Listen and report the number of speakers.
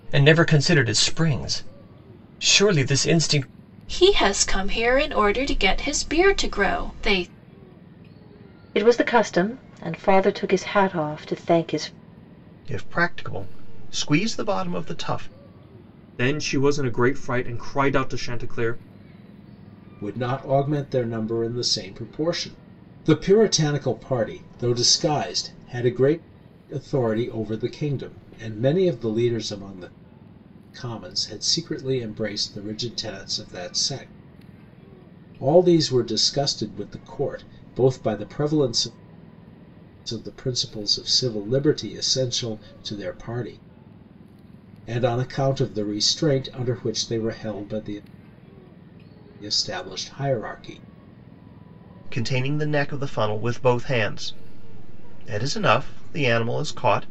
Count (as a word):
six